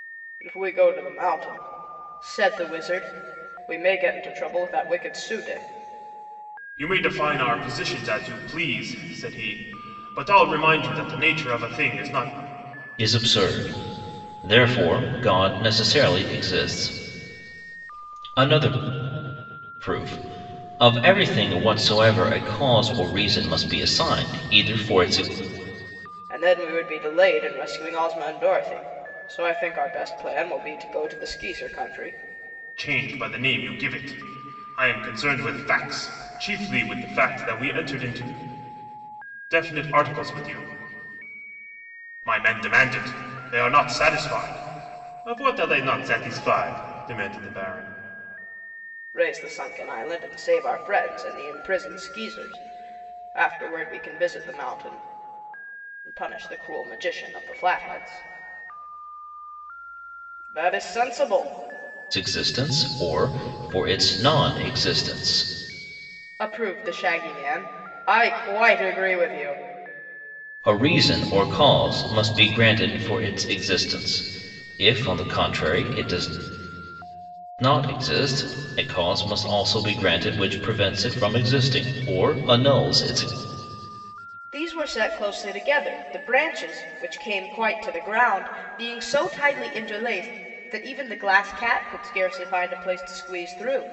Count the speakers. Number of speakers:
3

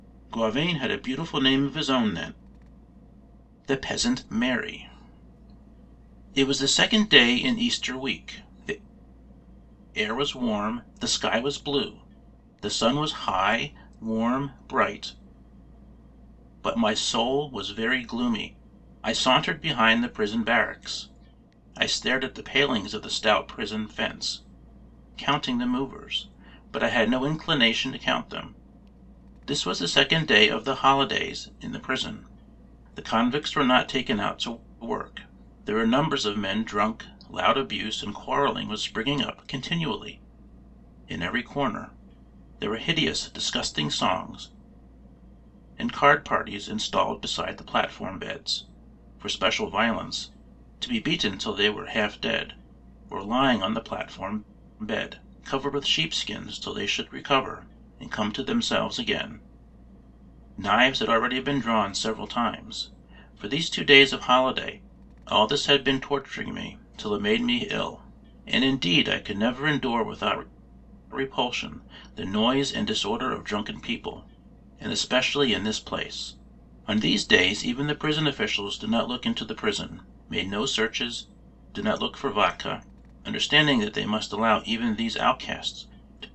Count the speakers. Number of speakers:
1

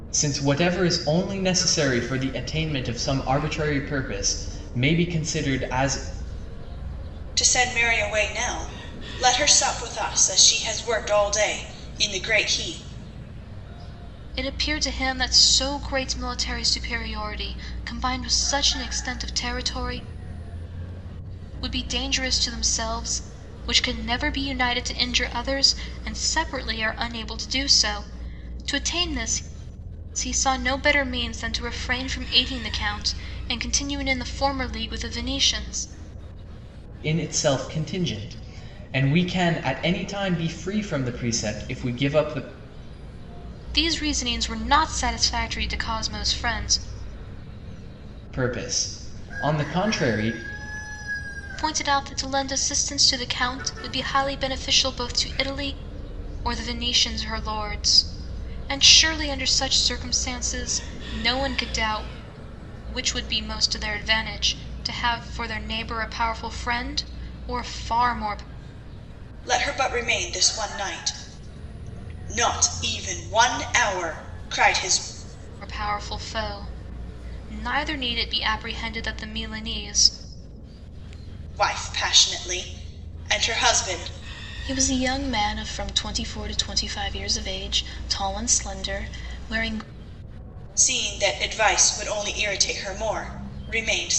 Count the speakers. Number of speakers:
3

